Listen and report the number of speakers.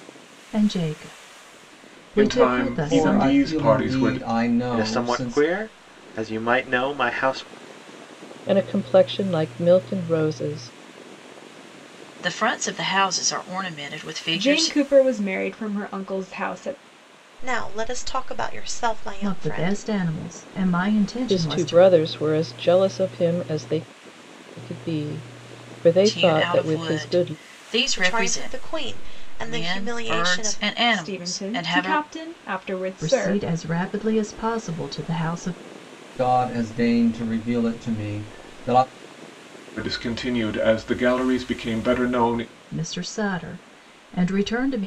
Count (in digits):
8